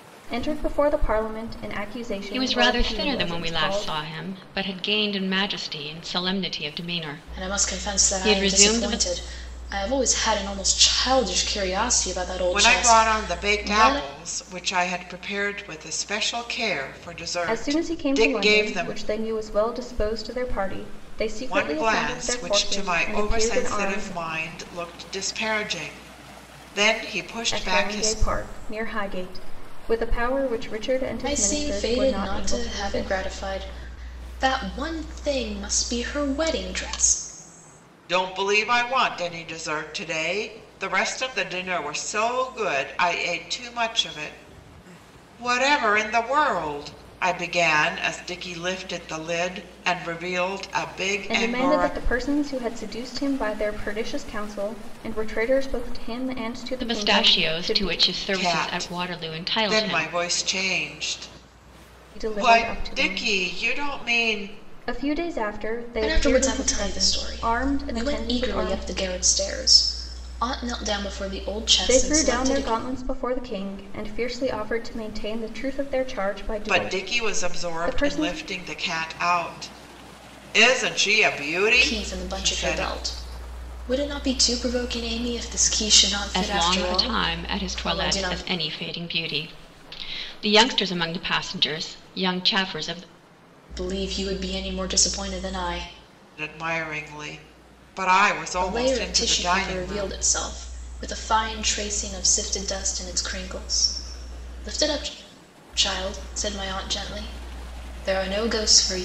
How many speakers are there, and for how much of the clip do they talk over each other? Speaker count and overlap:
4, about 26%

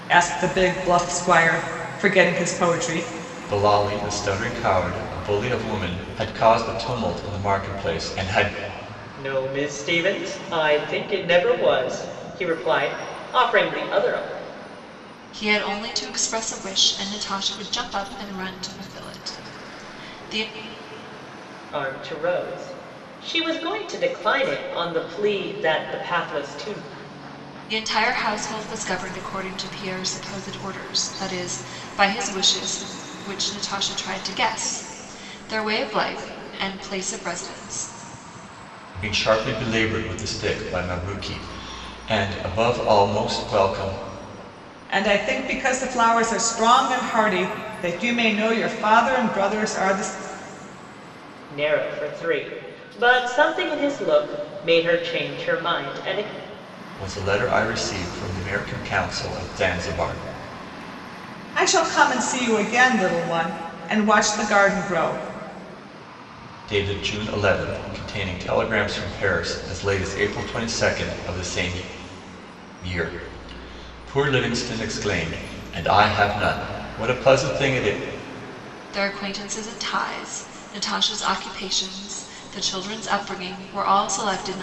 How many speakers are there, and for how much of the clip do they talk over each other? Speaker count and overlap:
4, no overlap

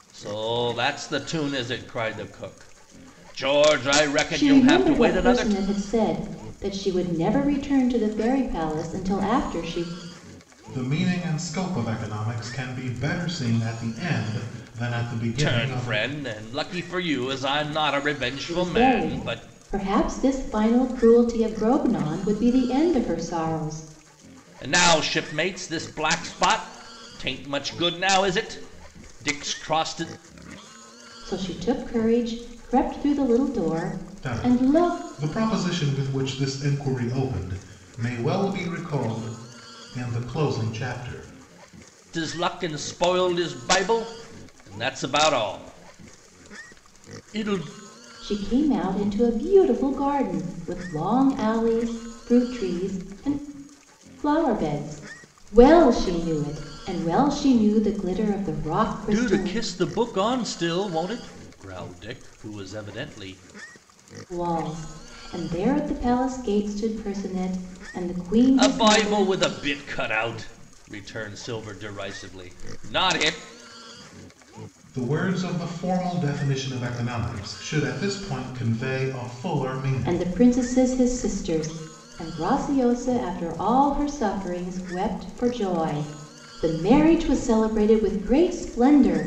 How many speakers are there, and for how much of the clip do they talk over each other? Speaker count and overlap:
3, about 6%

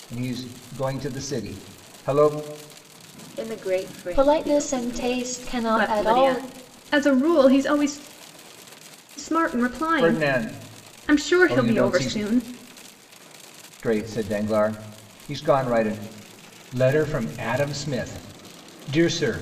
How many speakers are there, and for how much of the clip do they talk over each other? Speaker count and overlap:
4, about 19%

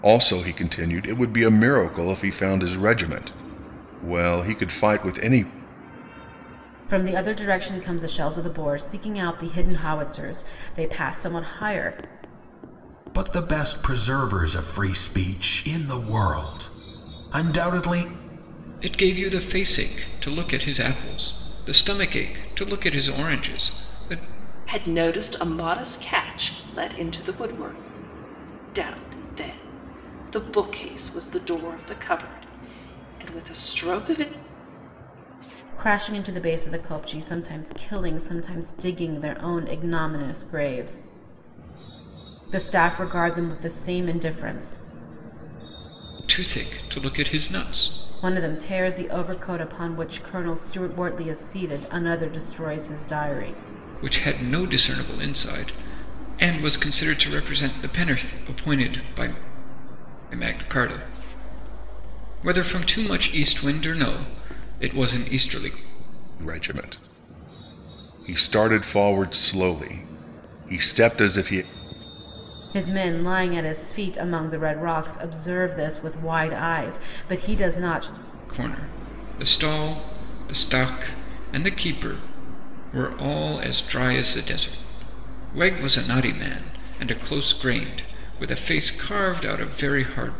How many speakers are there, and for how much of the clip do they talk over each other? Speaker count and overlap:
5, no overlap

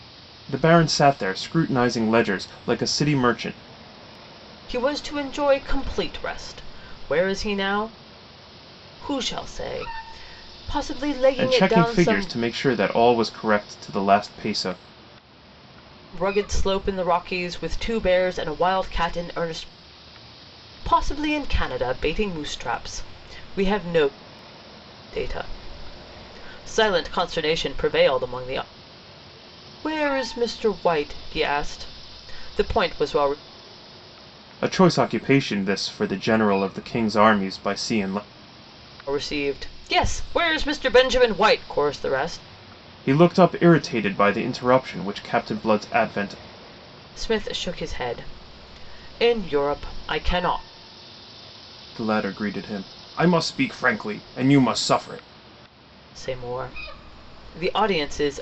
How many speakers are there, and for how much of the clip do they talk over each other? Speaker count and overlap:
2, about 2%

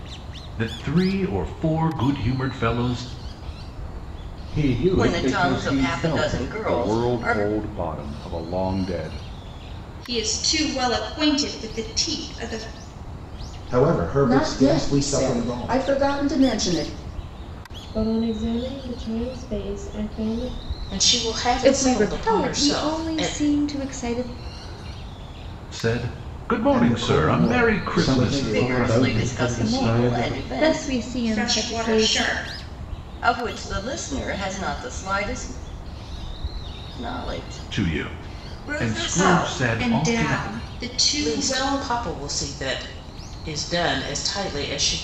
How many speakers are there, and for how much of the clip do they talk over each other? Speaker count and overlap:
10, about 32%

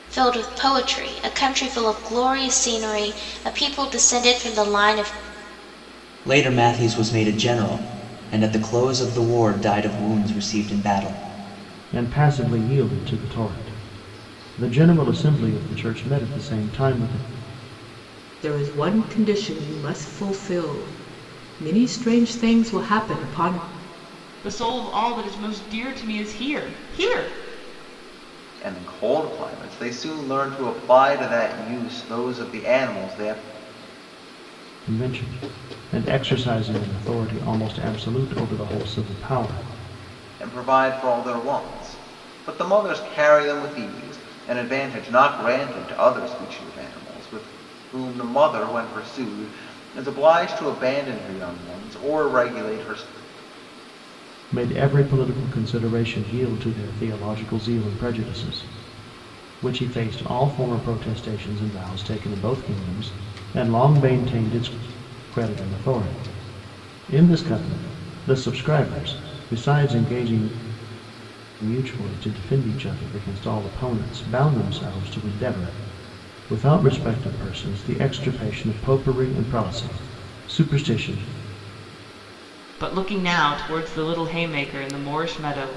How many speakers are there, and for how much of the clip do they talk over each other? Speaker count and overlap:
6, no overlap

